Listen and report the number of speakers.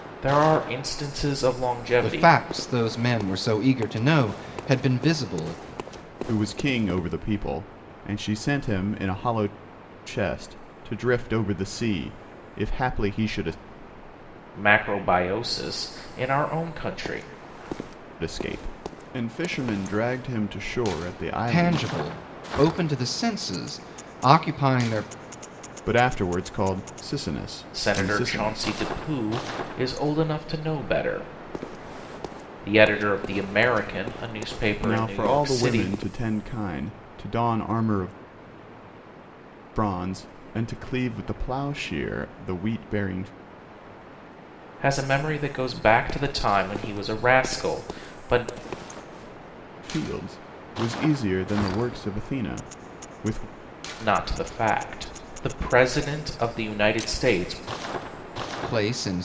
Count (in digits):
3